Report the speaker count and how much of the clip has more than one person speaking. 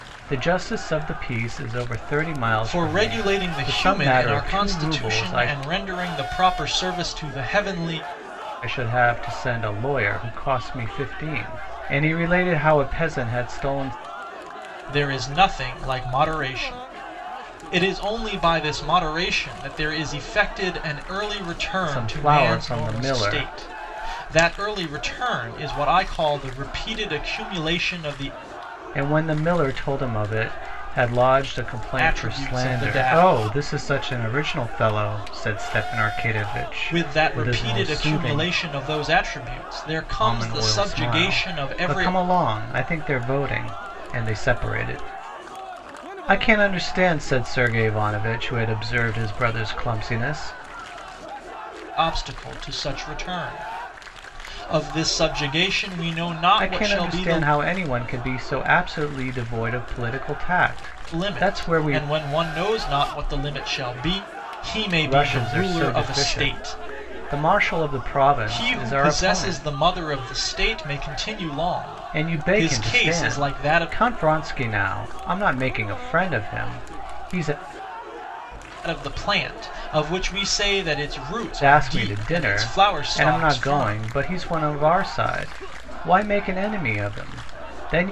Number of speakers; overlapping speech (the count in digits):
2, about 21%